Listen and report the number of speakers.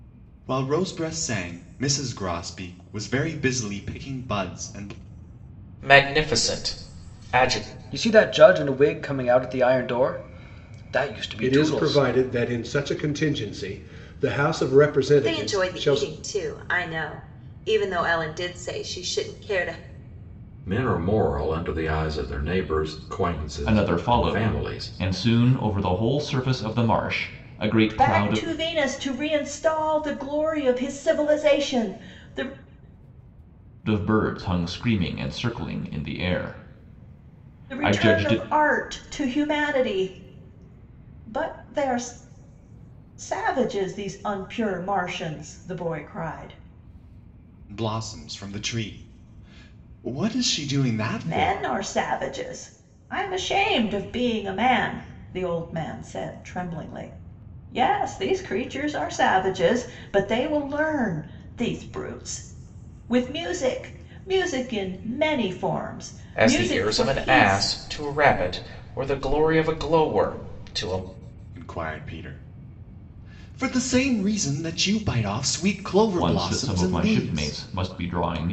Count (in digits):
8